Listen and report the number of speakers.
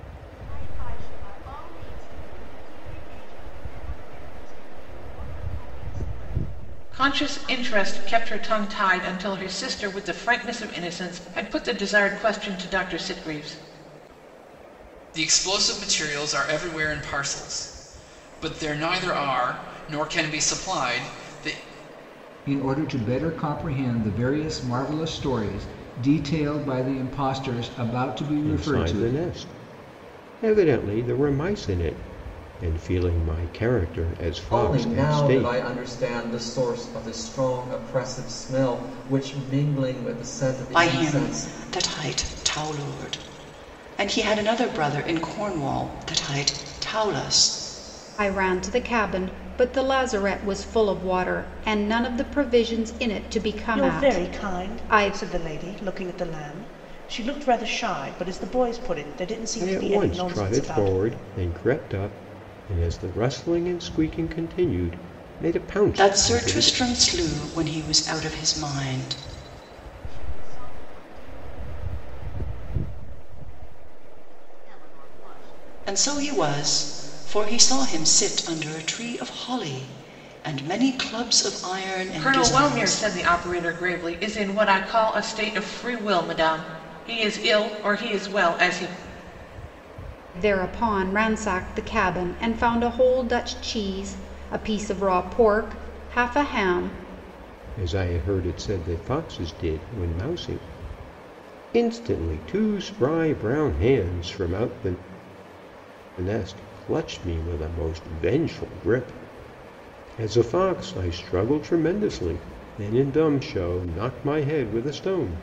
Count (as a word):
nine